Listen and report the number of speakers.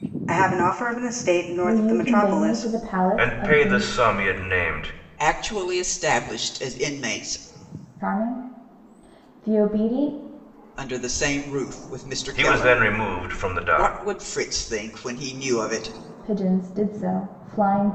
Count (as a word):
four